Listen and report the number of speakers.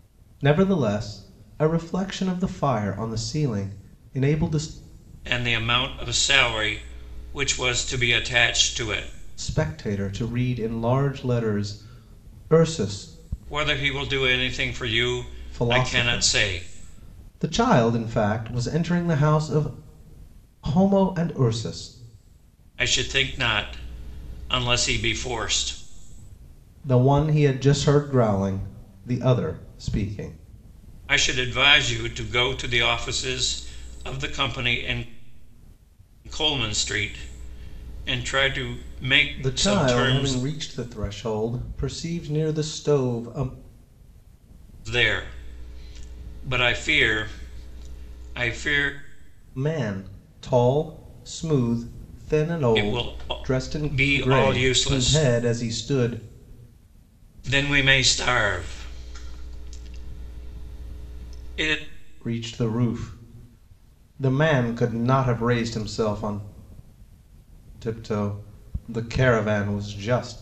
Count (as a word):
two